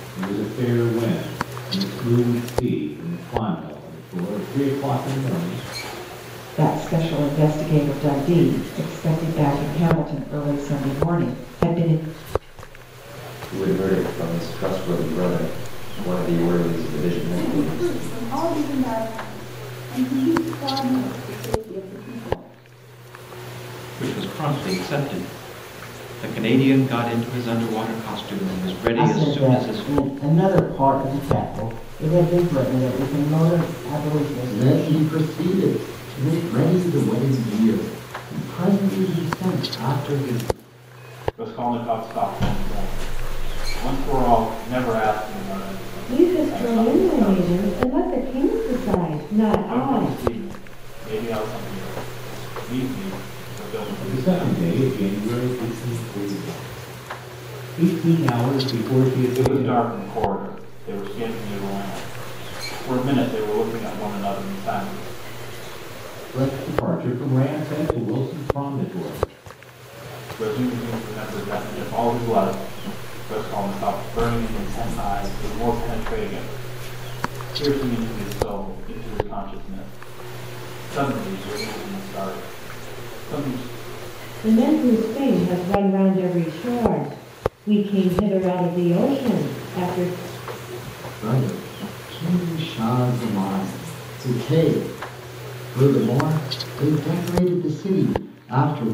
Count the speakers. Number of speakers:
nine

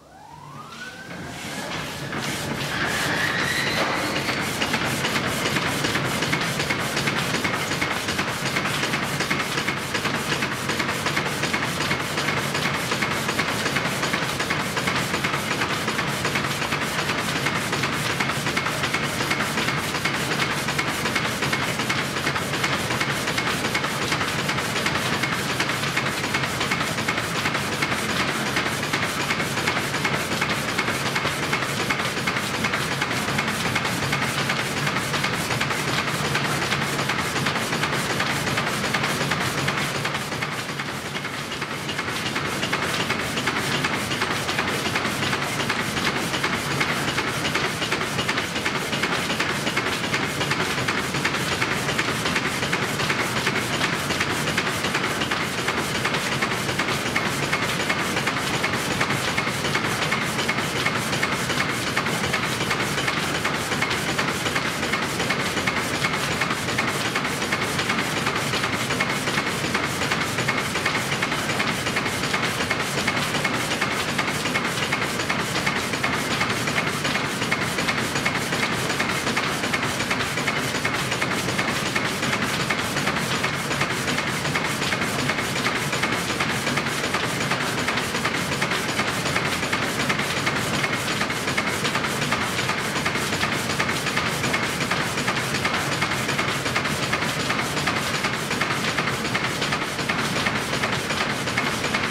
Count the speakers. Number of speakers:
zero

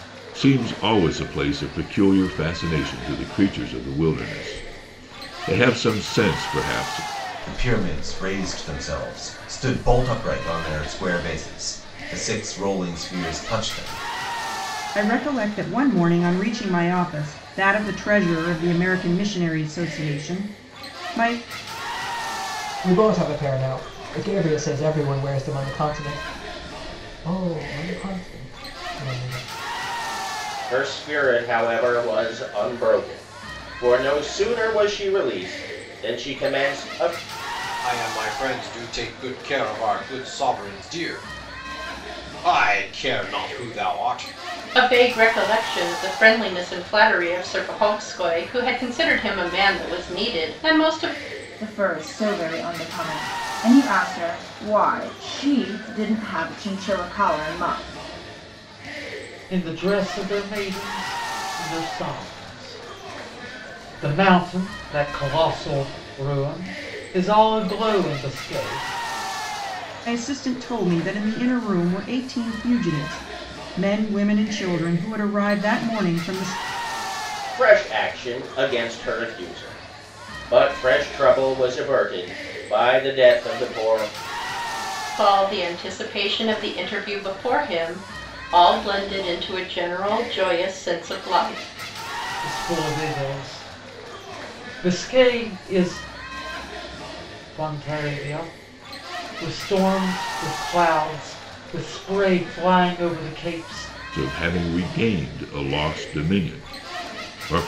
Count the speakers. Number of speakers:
nine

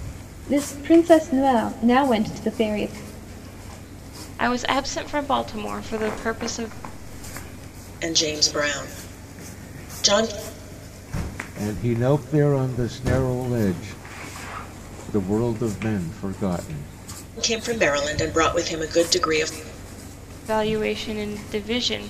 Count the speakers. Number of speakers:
four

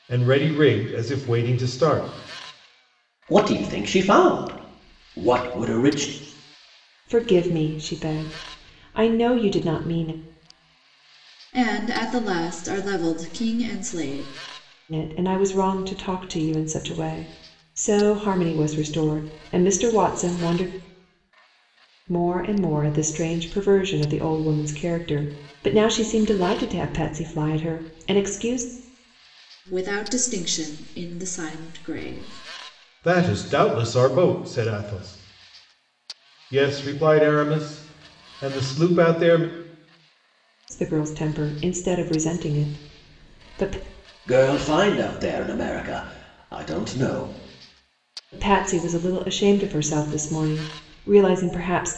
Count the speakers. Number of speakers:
four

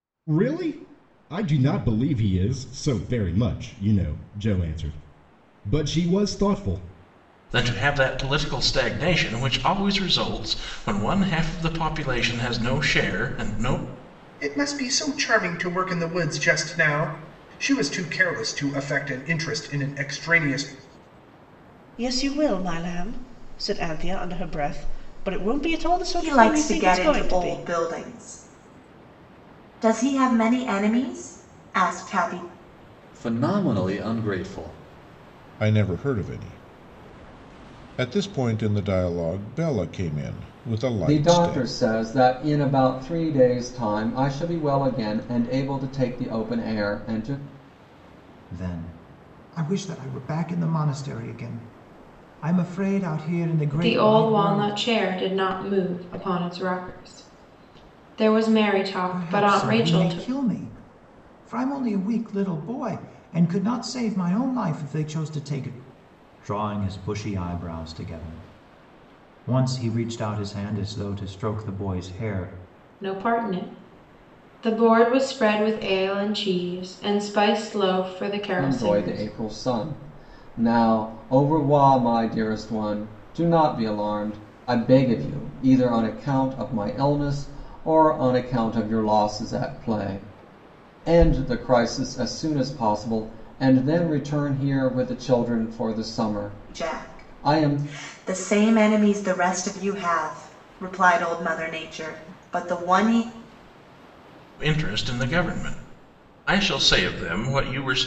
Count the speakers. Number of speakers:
ten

